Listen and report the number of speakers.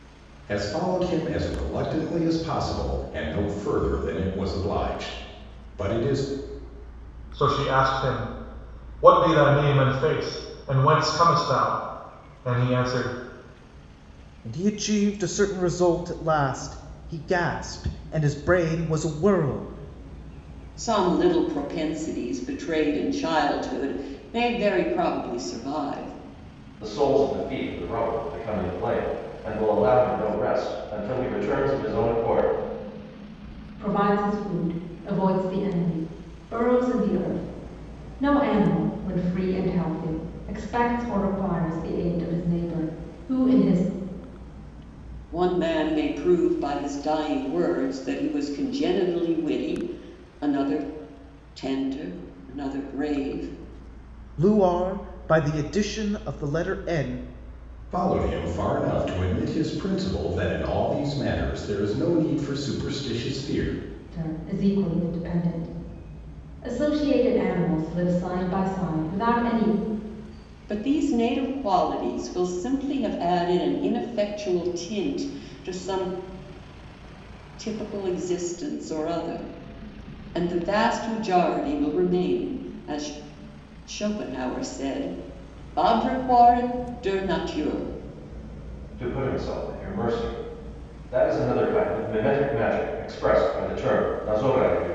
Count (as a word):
six